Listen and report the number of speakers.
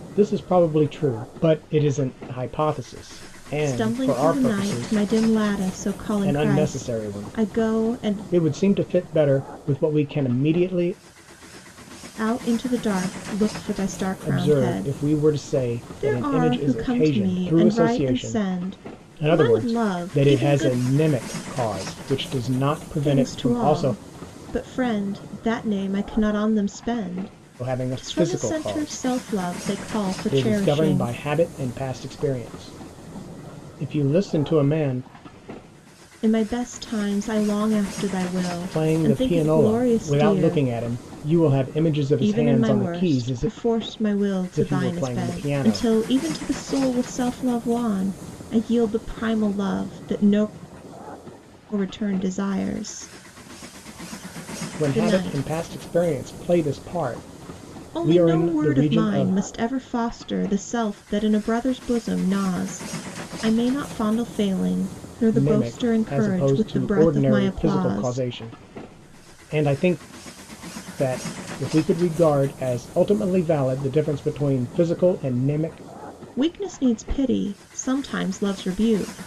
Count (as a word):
two